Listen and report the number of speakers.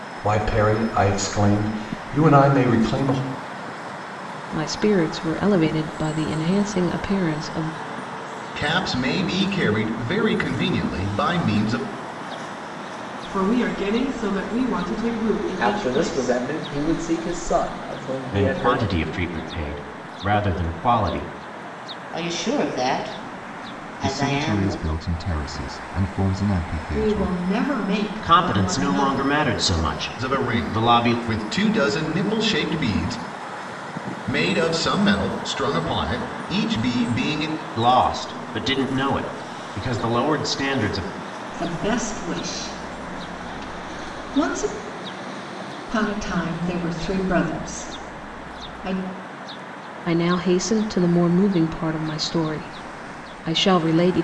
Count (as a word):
nine